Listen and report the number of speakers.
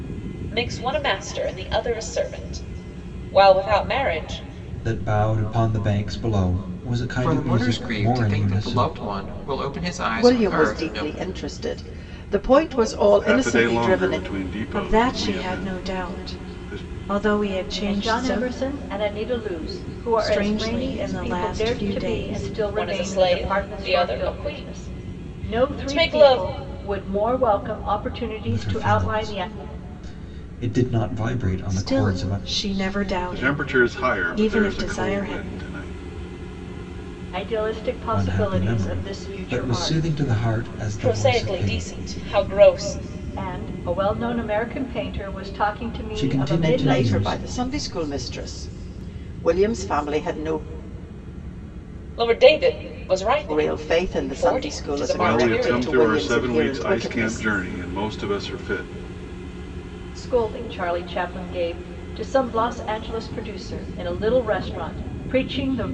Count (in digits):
7